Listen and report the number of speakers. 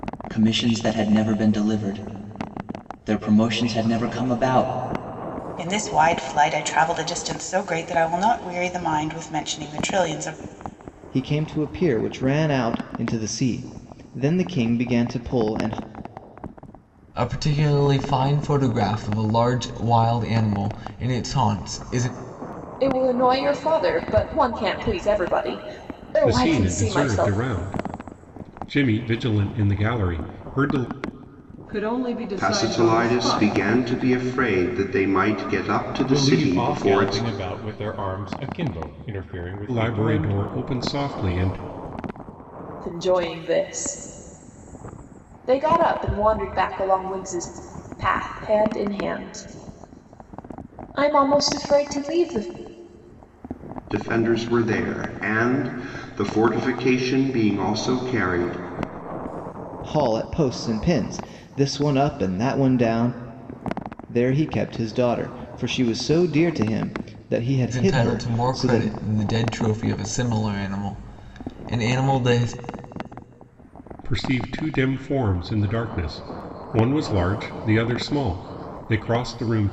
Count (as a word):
nine